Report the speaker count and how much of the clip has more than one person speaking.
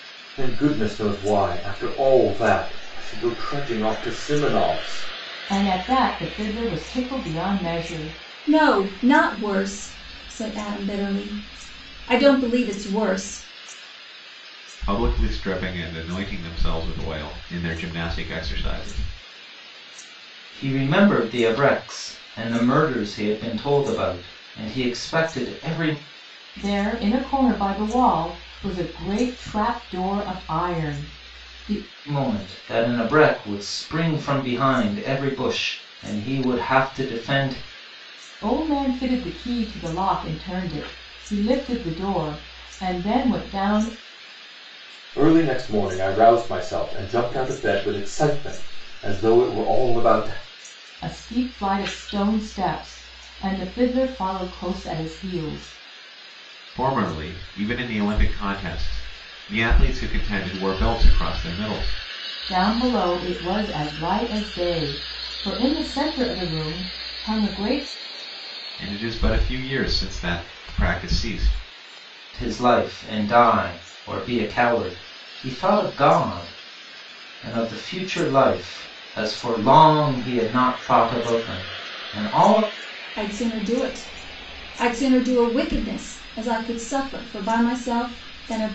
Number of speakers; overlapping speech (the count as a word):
five, no overlap